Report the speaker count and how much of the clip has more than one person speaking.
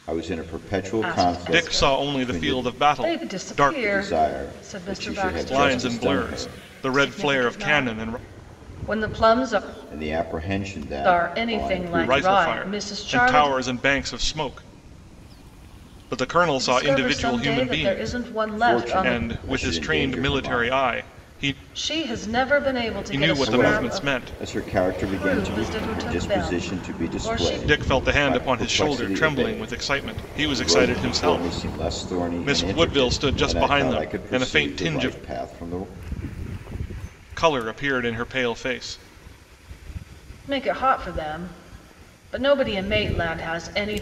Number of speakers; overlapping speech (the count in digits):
3, about 56%